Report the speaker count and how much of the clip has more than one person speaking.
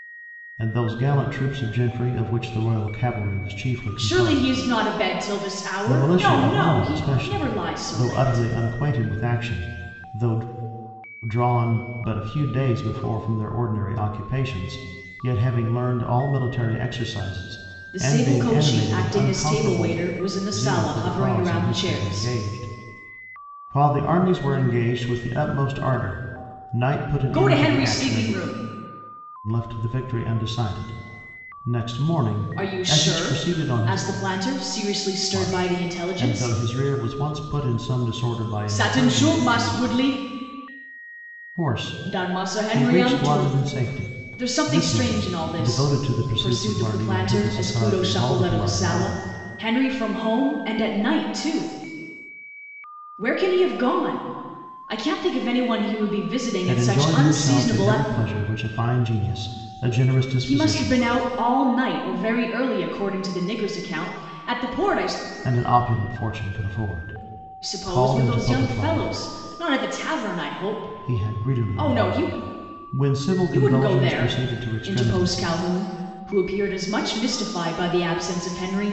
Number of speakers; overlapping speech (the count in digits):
2, about 33%